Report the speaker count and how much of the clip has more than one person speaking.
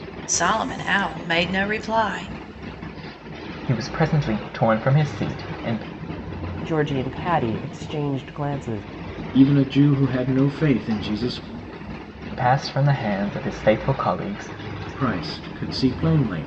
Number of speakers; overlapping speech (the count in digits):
4, no overlap